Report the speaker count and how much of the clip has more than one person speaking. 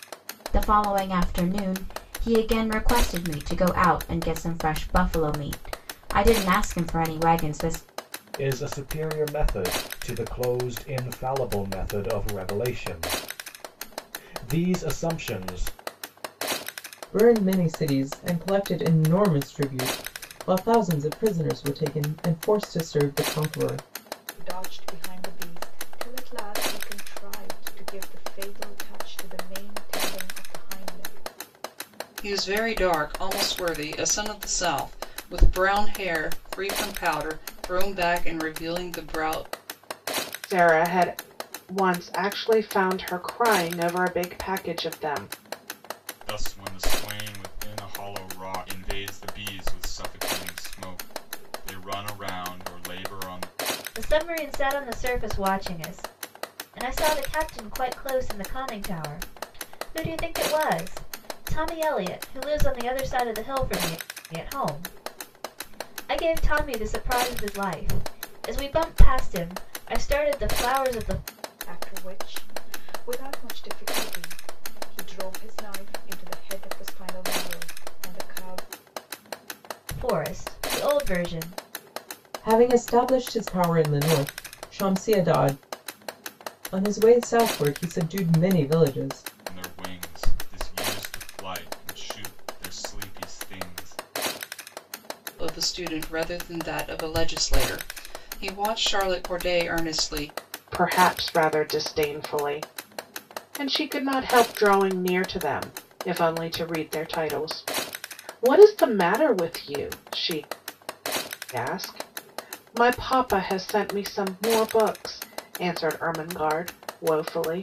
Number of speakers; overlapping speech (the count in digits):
8, no overlap